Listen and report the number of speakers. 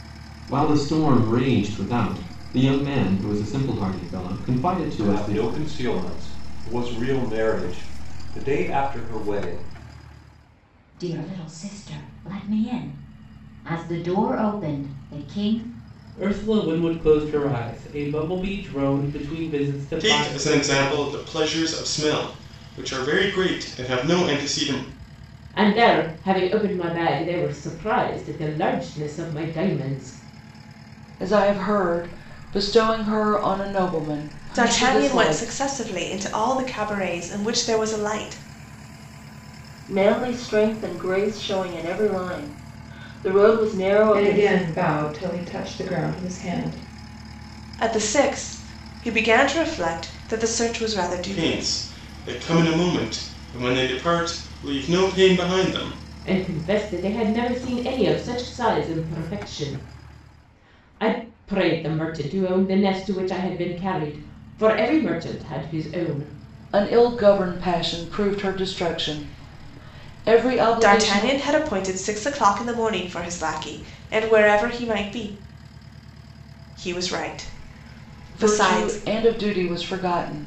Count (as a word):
ten